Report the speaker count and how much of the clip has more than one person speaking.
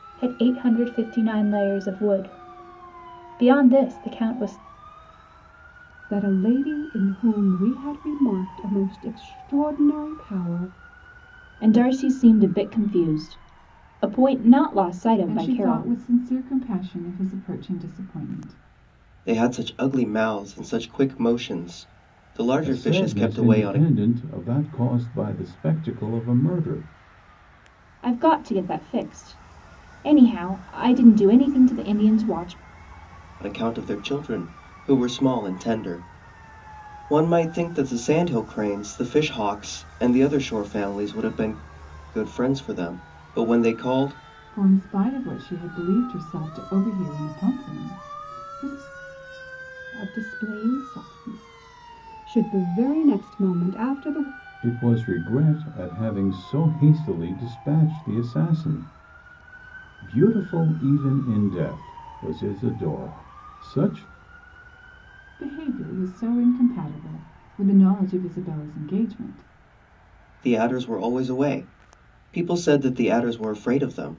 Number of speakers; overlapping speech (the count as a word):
six, about 3%